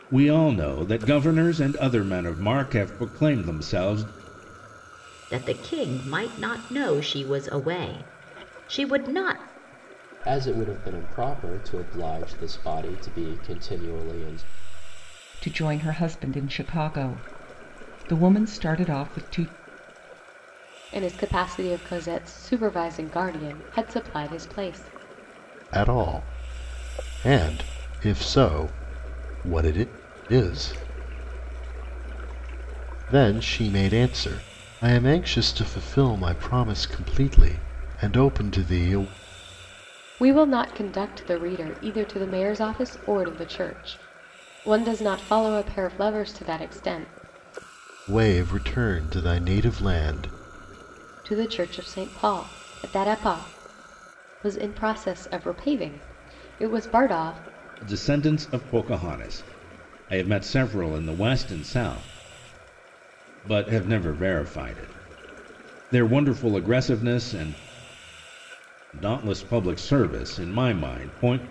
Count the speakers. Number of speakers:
six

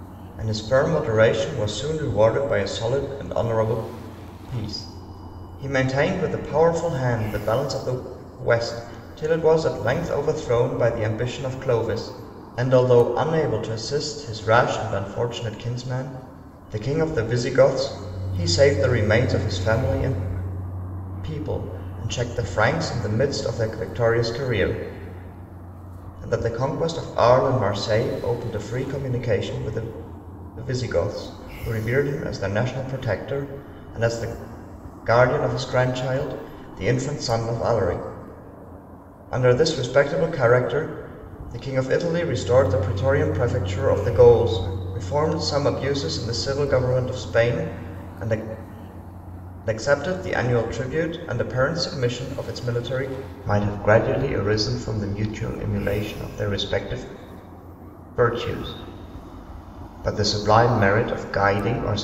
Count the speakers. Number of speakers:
one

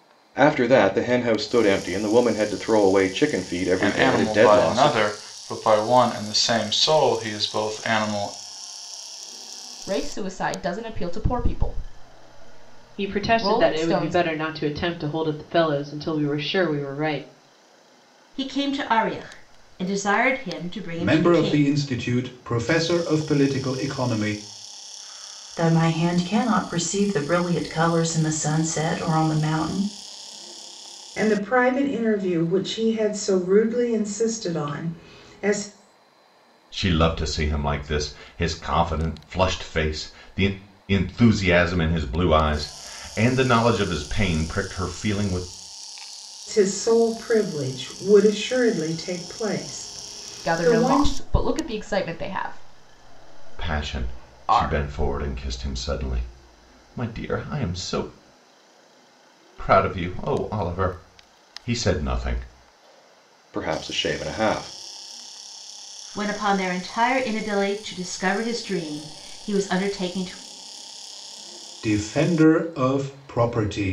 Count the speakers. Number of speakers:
nine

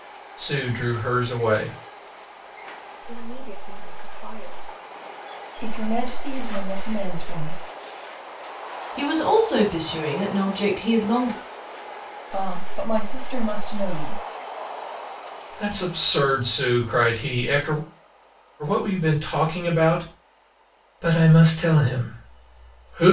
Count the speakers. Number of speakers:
four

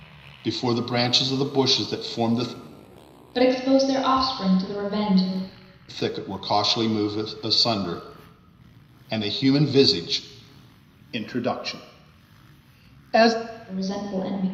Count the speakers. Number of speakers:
two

